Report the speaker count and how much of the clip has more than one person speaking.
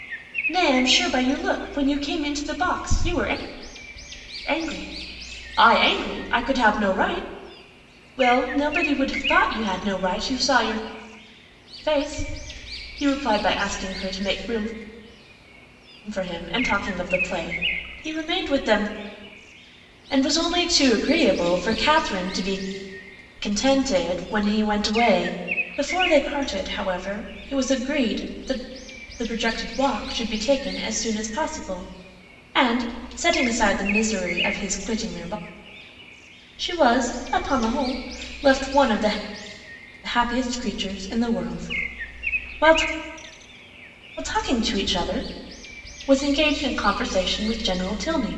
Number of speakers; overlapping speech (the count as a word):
one, no overlap